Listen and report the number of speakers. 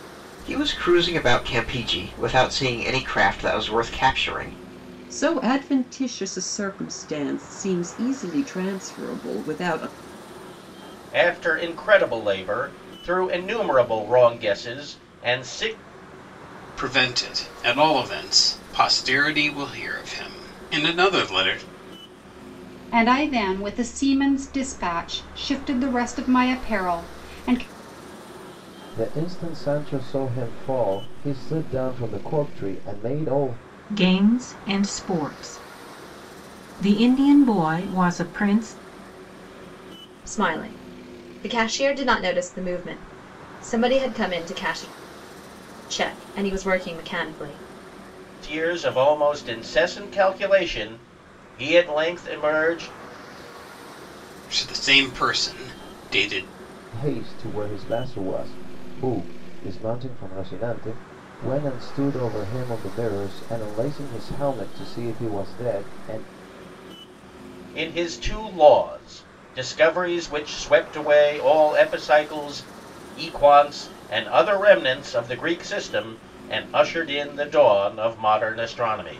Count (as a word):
eight